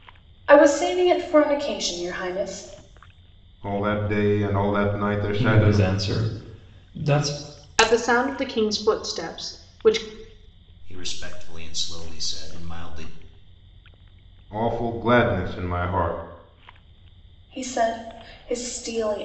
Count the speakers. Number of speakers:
5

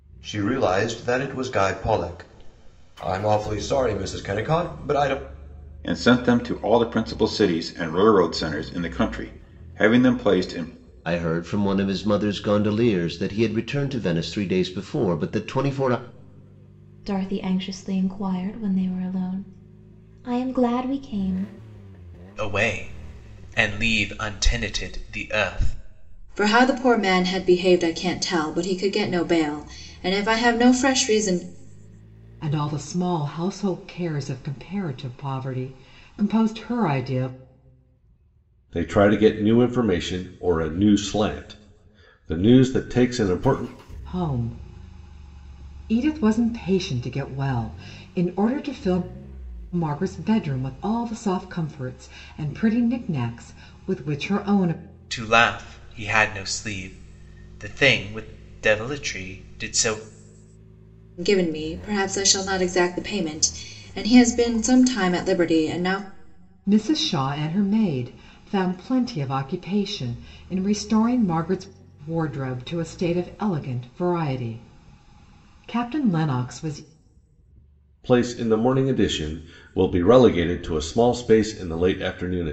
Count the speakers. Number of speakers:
8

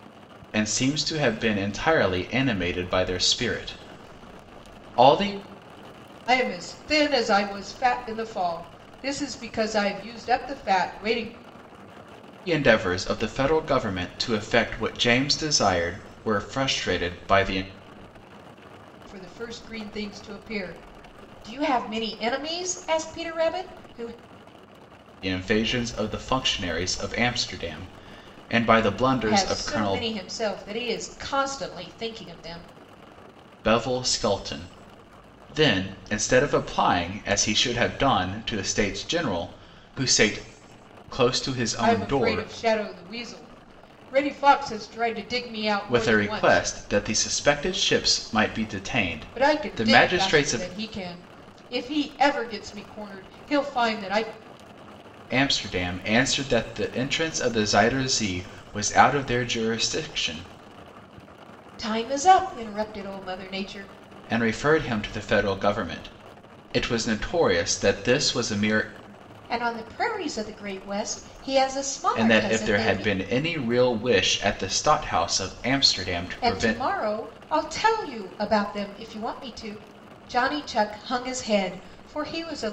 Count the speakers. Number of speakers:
2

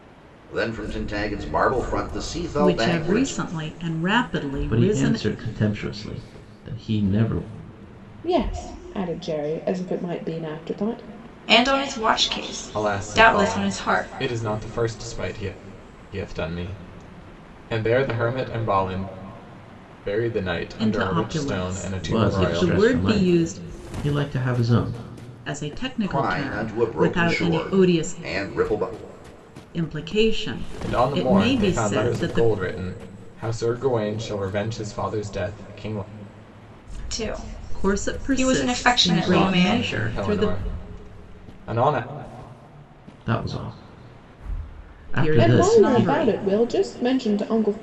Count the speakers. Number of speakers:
6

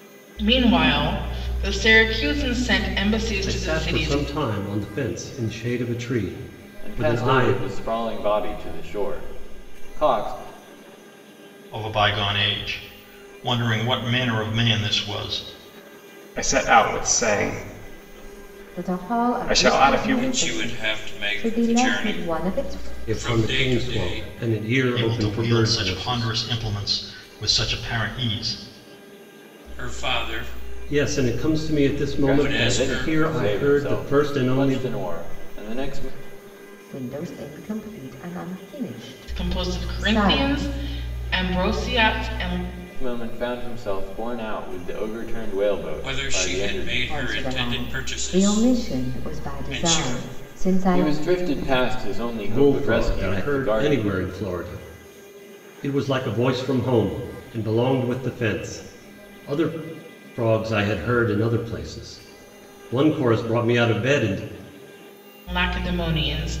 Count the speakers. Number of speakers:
7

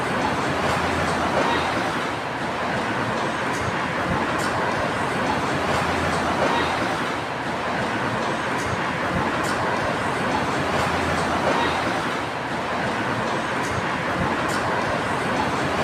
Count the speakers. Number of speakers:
0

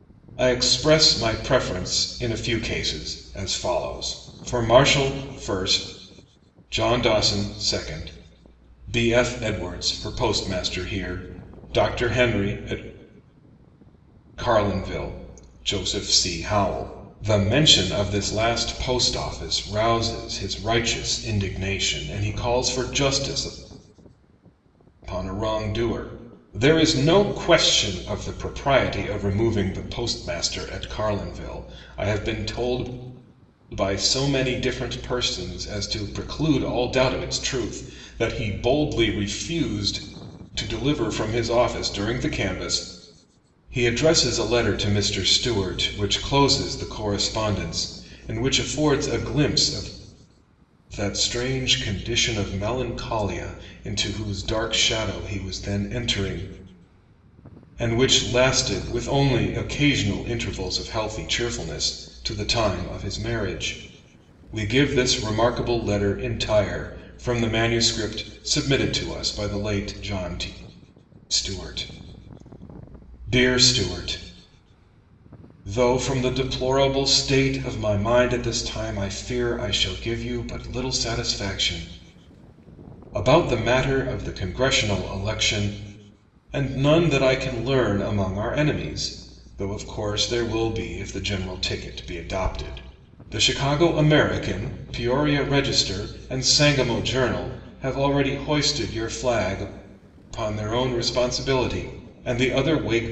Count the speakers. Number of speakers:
1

